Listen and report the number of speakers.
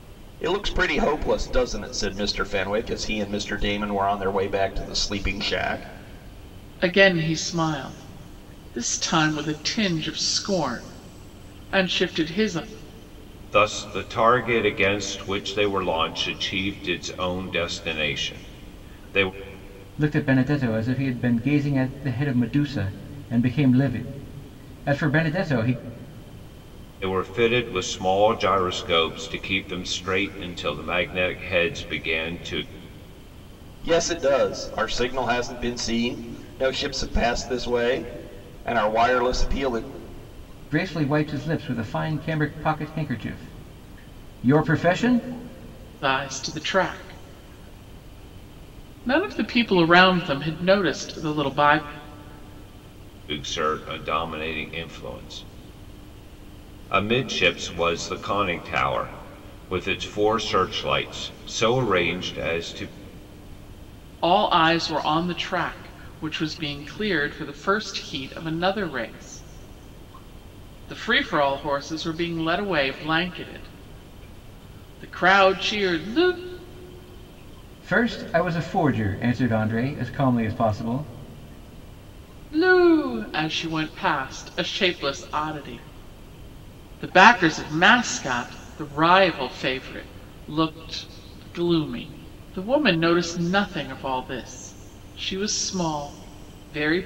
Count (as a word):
four